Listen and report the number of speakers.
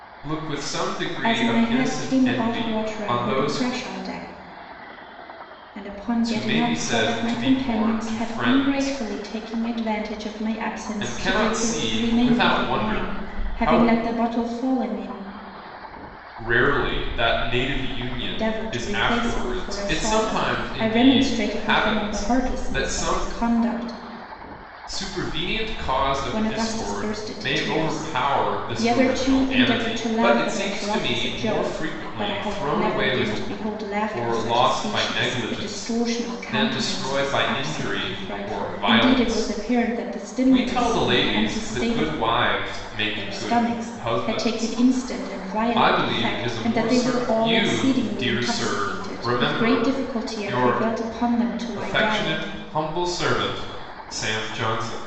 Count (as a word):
two